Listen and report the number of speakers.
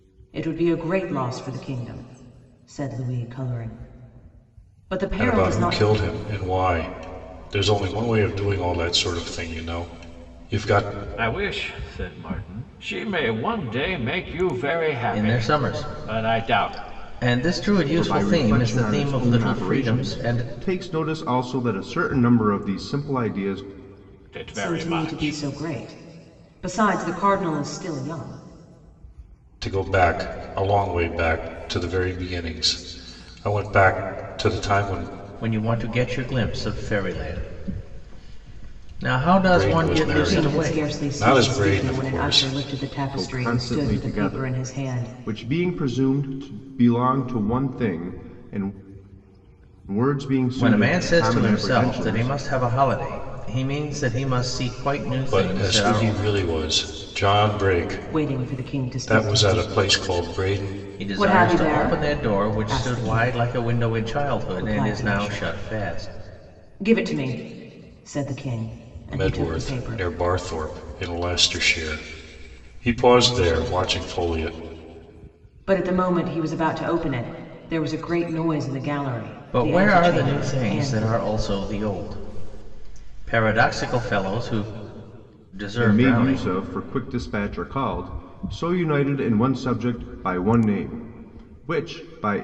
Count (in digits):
5